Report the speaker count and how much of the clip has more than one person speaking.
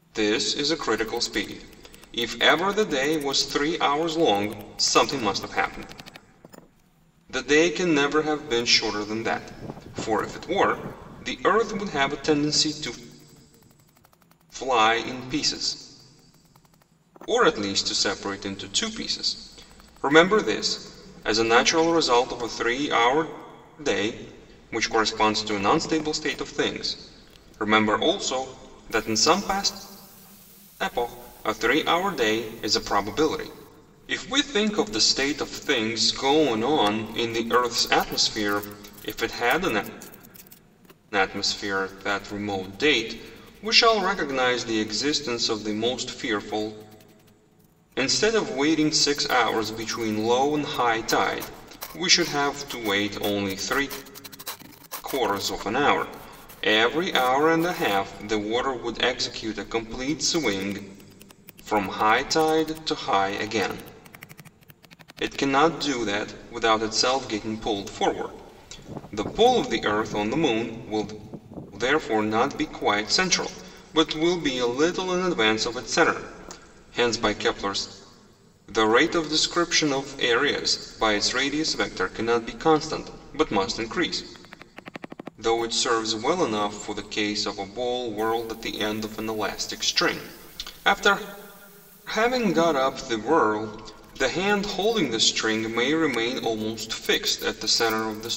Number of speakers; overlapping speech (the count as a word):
one, no overlap